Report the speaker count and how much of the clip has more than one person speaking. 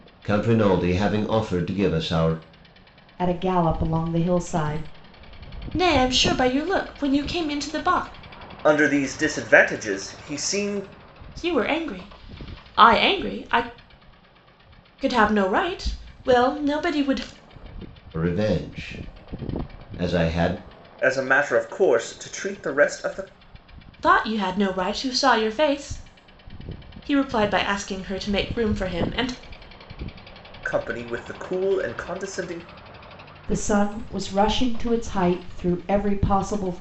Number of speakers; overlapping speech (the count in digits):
4, no overlap